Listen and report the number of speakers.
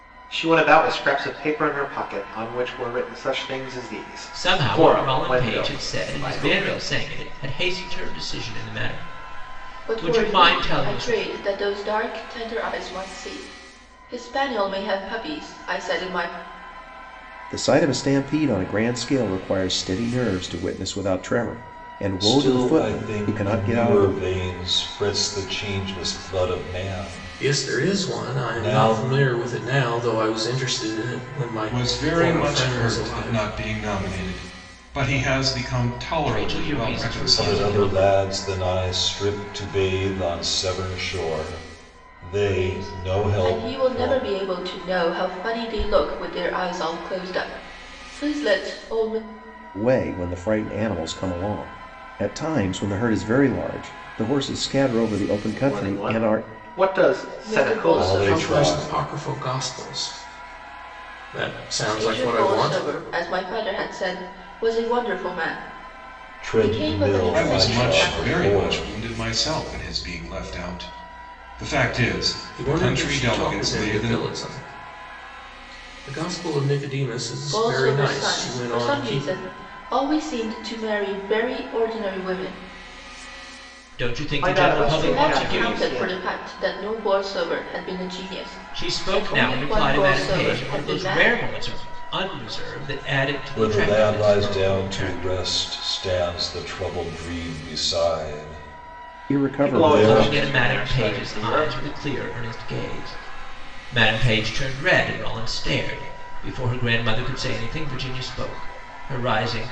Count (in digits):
7